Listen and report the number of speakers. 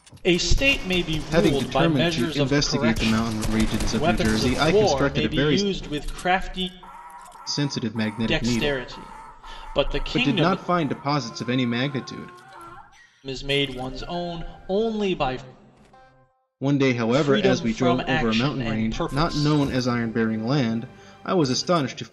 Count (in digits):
2